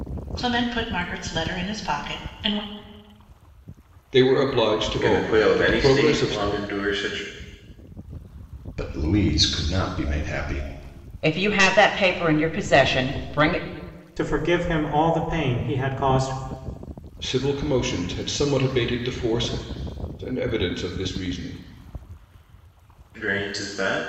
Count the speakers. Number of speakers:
6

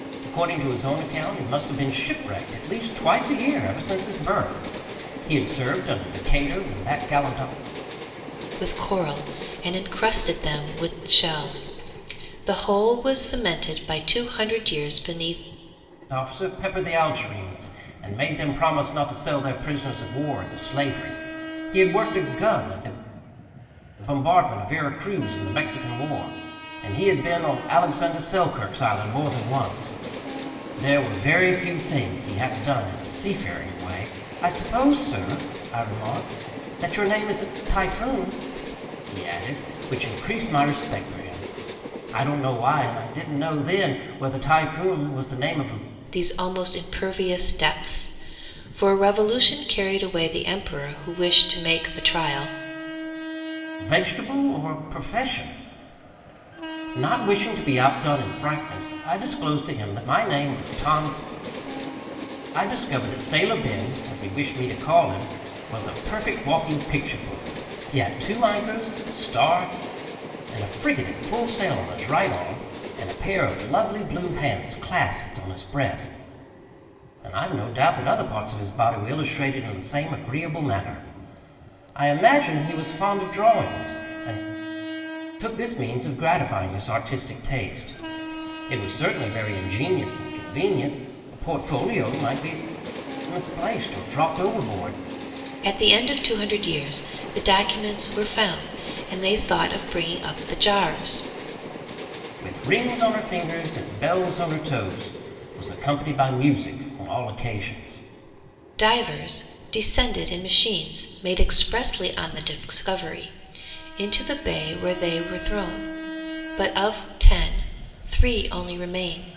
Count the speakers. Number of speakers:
2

